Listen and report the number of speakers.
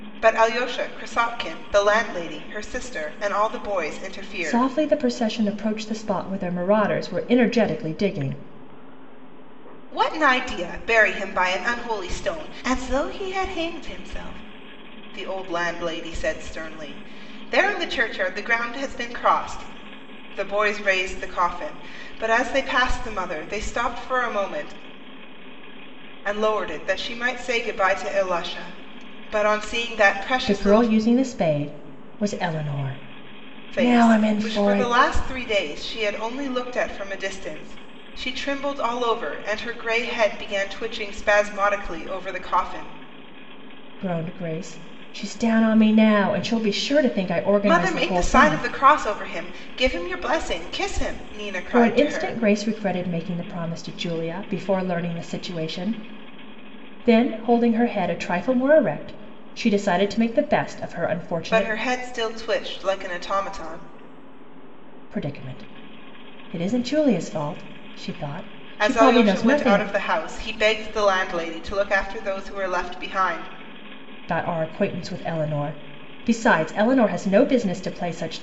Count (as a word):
two